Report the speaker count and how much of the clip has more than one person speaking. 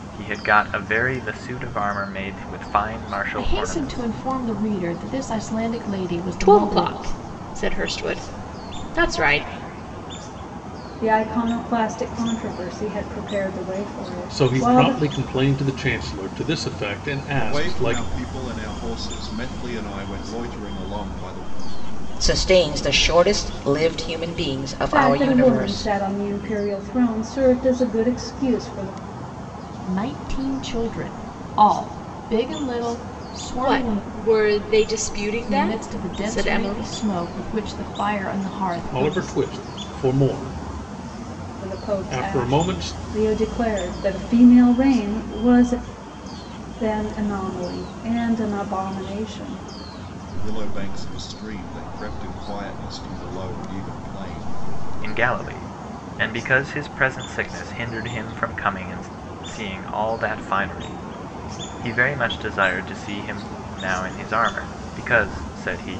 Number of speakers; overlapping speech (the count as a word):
seven, about 12%